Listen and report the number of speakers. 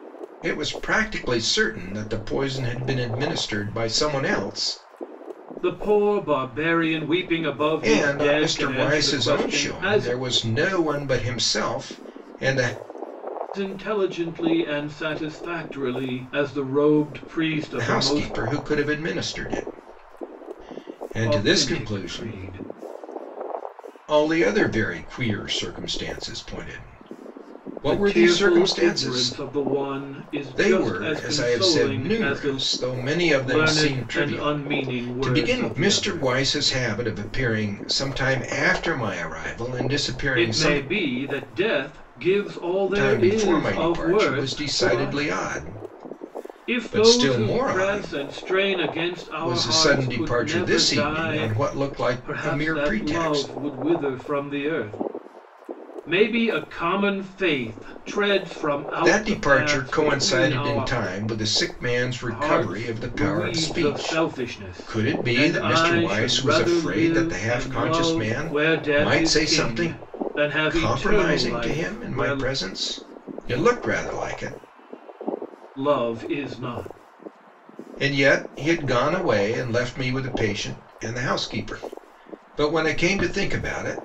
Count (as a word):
two